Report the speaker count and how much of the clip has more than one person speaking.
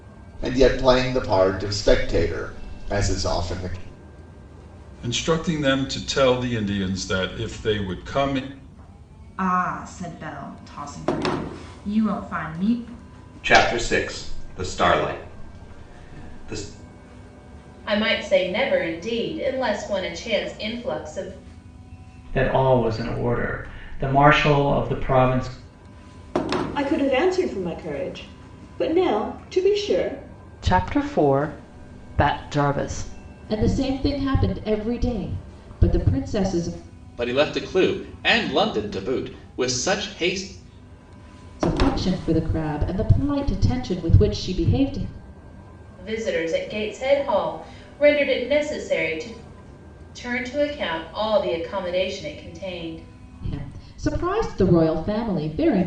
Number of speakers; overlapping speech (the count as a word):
ten, no overlap